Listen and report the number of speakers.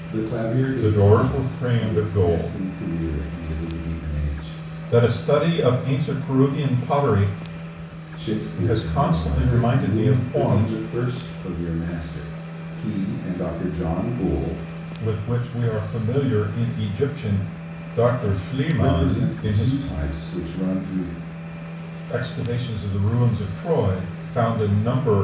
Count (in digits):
2